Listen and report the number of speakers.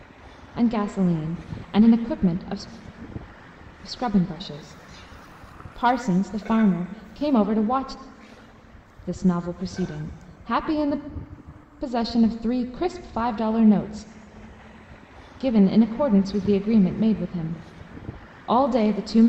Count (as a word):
one